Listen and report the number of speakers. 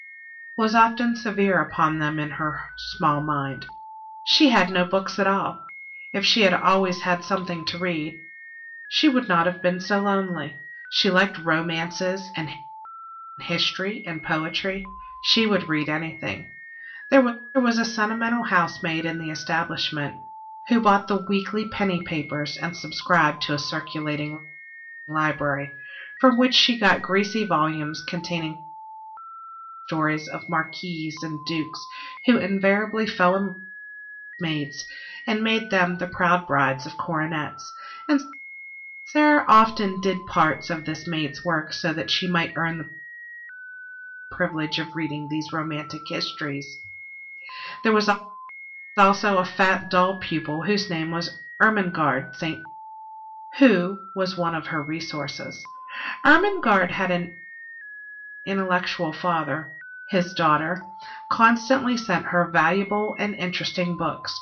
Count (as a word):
one